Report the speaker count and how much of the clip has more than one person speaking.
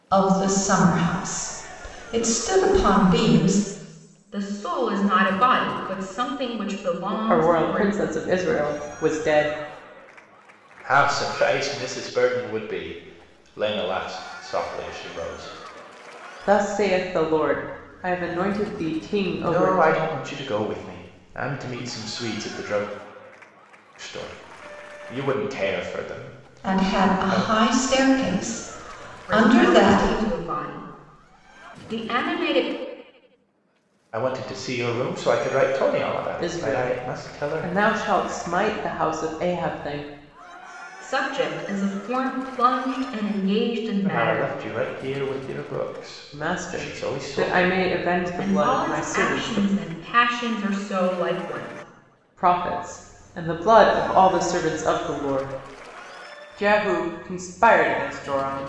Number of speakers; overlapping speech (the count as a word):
four, about 12%